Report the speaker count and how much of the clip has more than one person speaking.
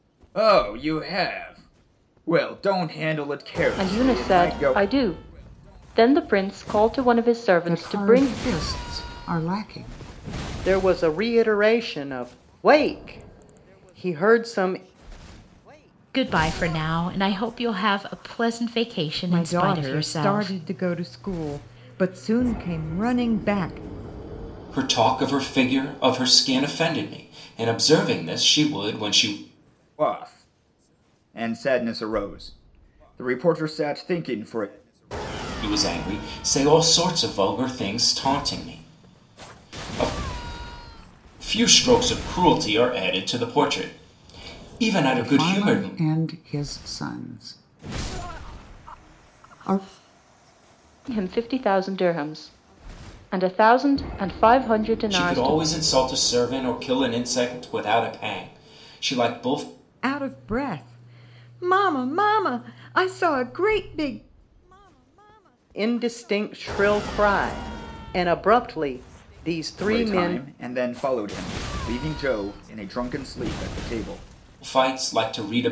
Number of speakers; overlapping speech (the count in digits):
7, about 7%